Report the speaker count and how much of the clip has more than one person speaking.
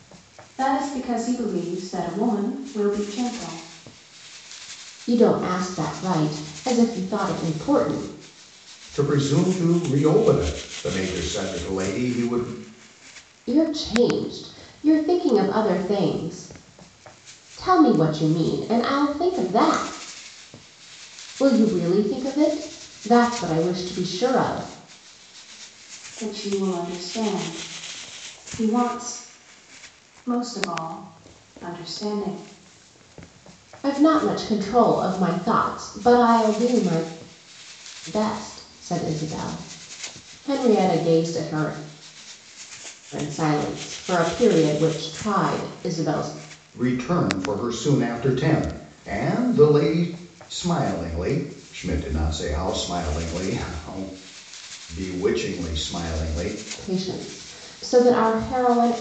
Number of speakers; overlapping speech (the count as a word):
three, no overlap